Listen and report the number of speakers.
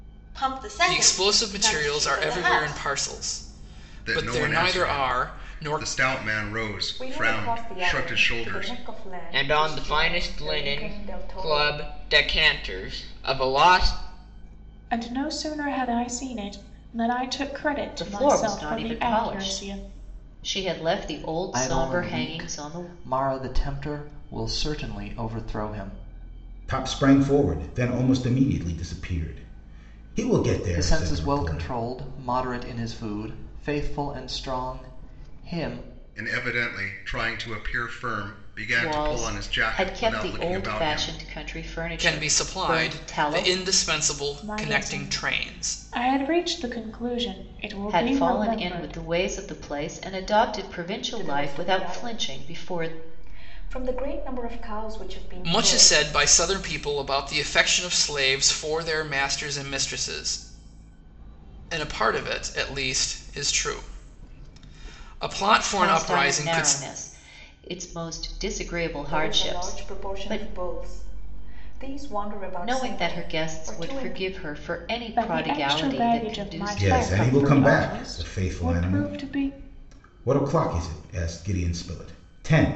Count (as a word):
nine